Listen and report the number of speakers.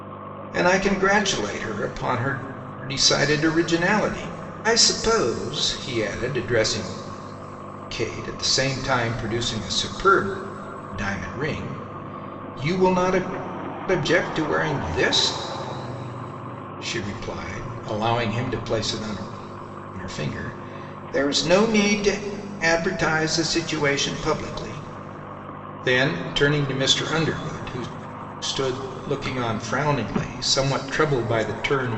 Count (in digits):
1